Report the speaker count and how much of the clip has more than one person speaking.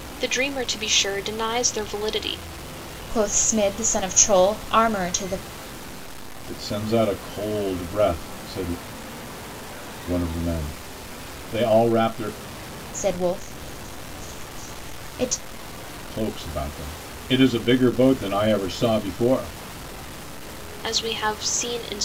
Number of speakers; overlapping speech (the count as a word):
three, no overlap